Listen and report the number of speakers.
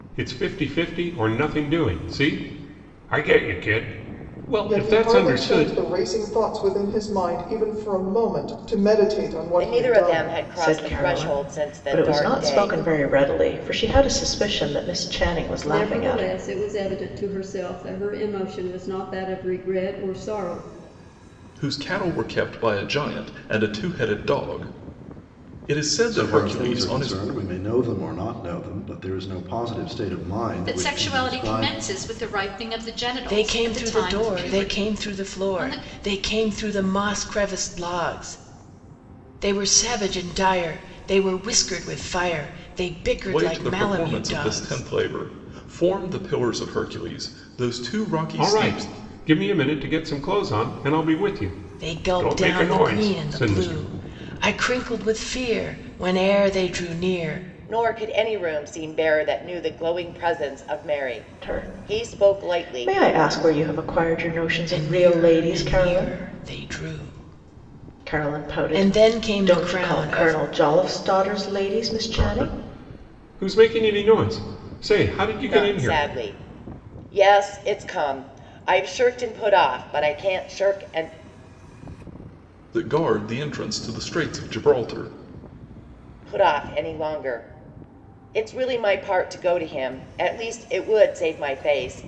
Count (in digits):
9